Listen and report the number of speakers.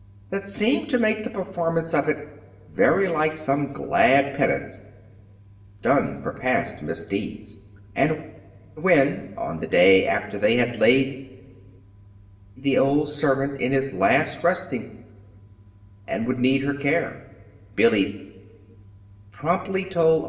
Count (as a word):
one